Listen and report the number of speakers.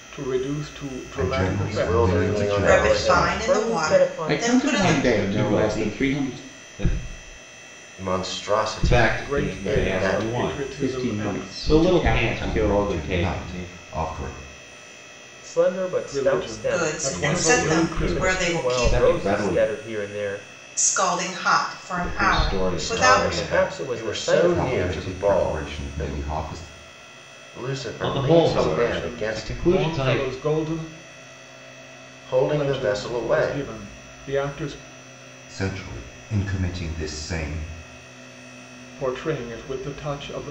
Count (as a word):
seven